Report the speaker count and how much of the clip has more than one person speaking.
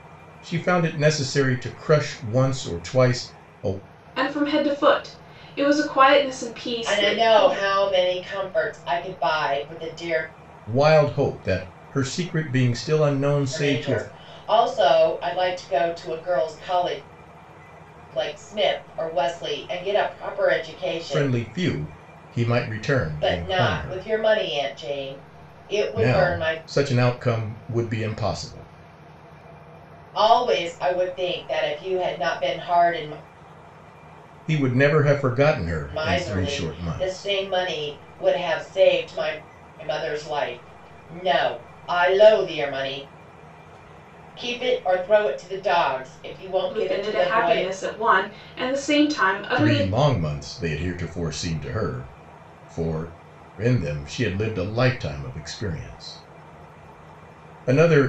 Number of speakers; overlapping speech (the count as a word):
three, about 10%